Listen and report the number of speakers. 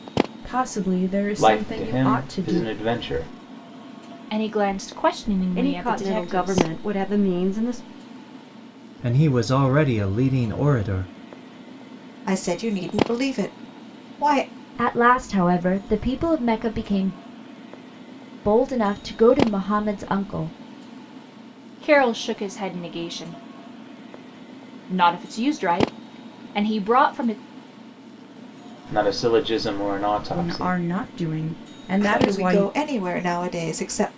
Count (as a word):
seven